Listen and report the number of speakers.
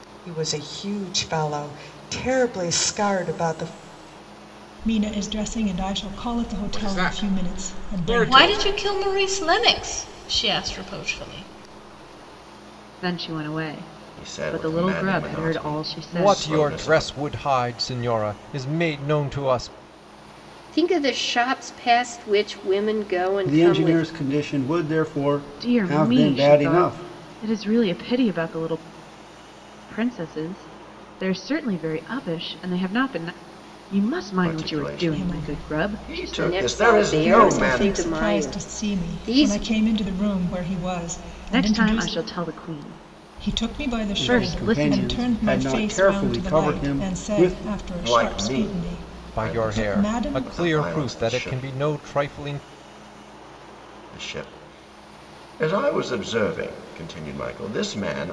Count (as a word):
nine